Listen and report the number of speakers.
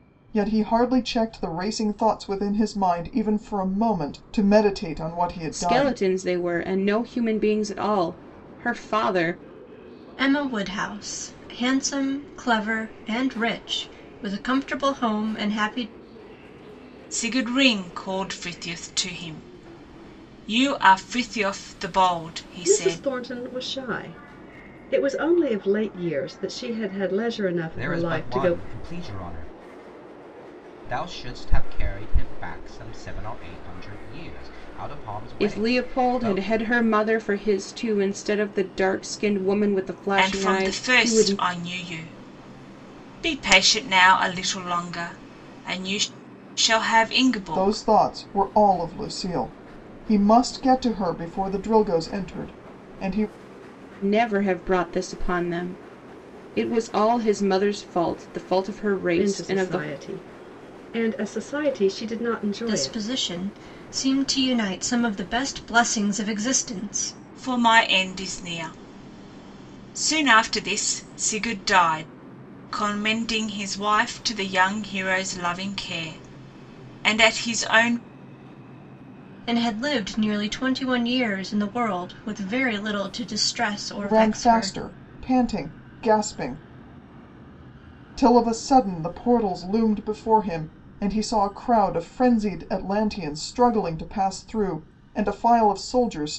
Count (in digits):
6